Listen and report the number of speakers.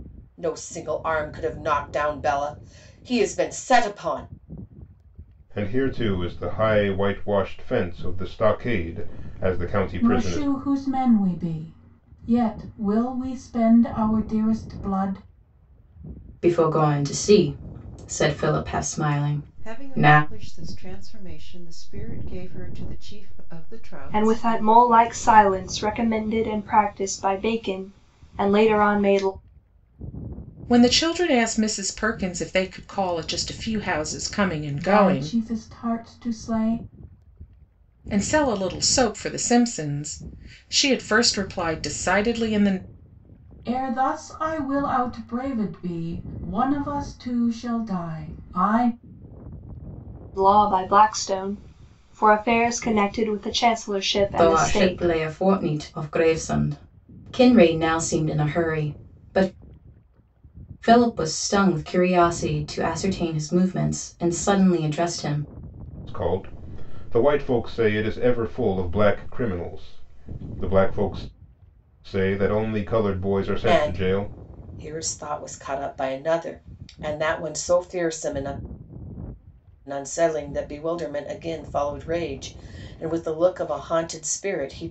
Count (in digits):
7